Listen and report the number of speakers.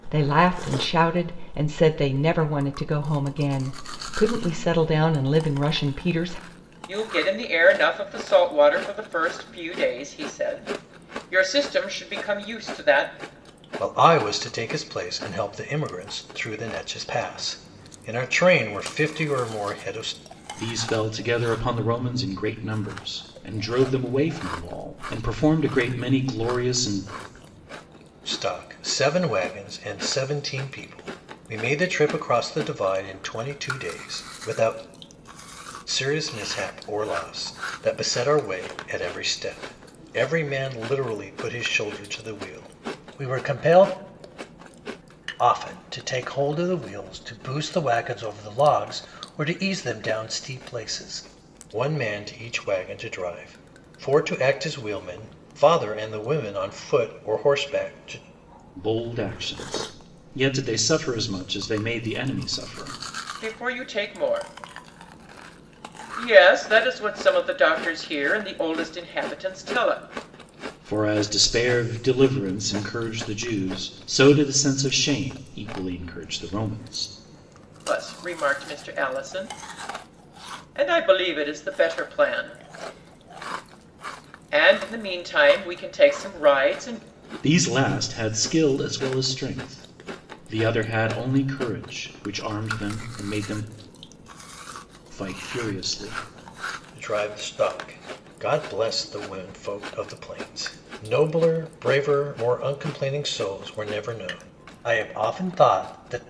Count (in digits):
4